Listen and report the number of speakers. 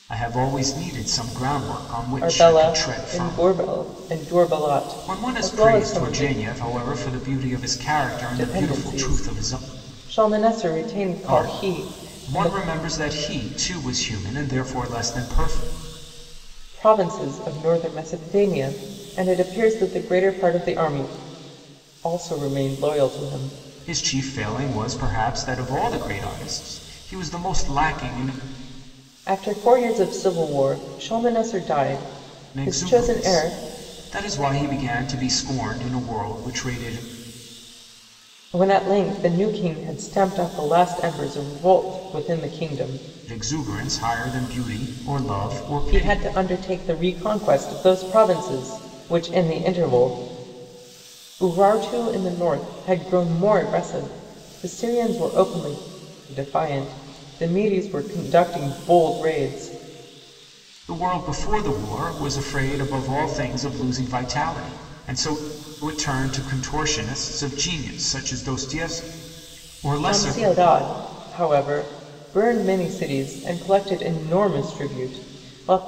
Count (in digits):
2